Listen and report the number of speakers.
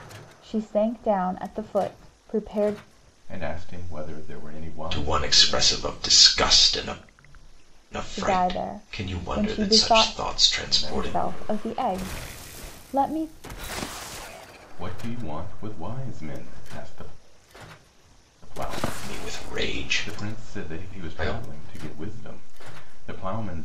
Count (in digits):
3